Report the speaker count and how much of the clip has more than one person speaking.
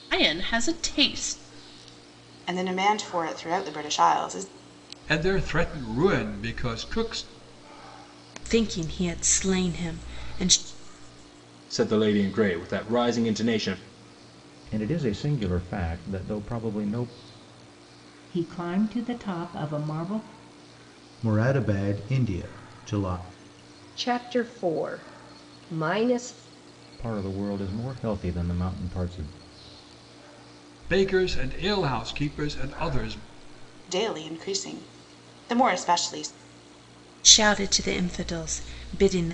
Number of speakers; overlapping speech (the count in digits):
9, no overlap